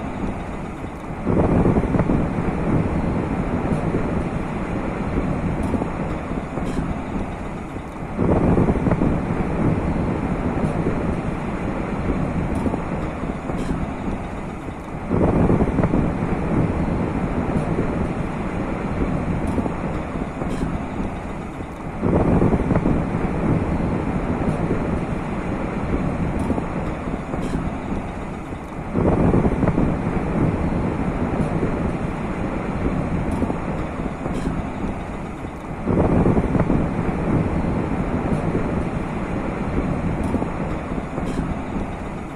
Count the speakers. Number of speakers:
0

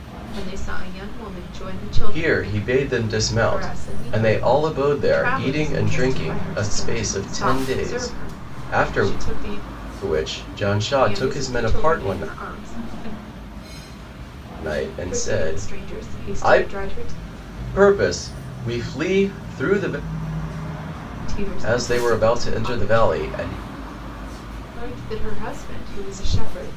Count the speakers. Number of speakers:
2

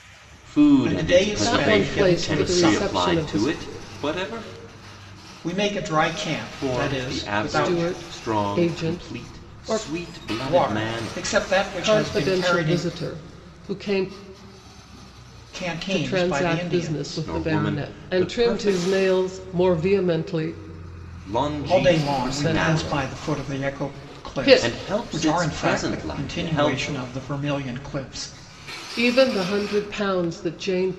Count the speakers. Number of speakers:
3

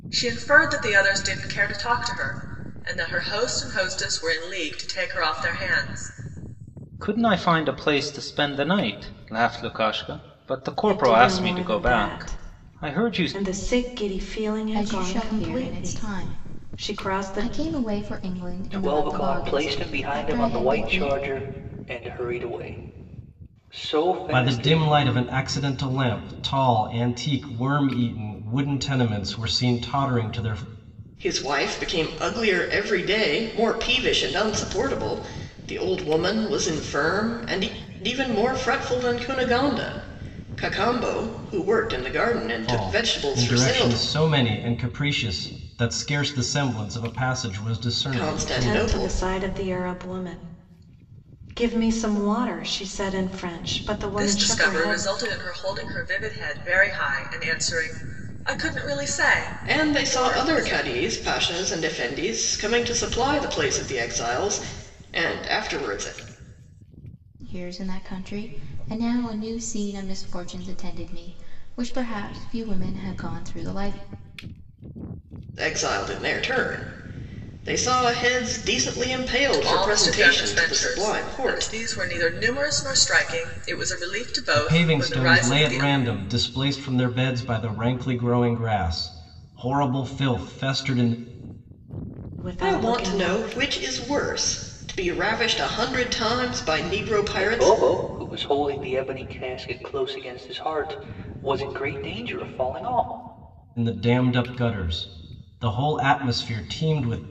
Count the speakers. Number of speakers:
7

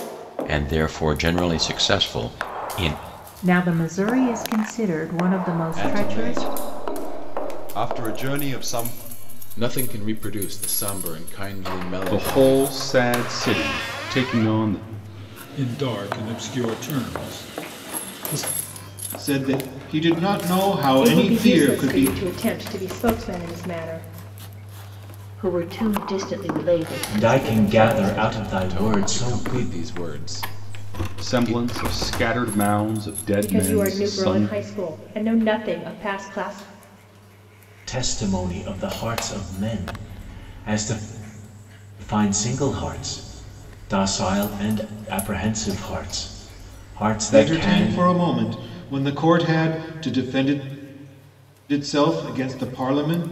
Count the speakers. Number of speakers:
10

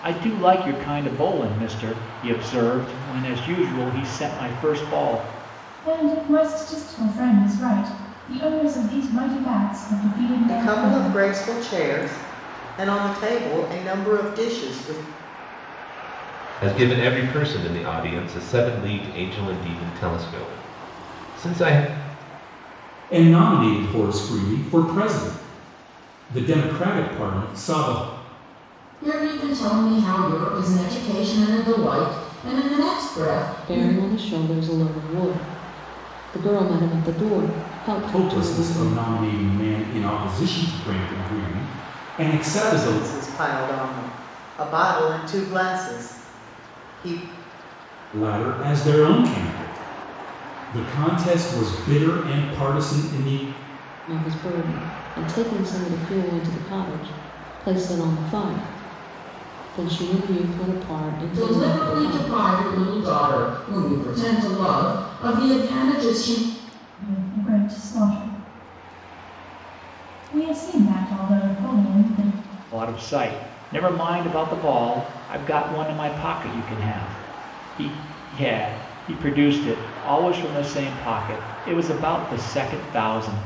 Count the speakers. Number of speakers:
7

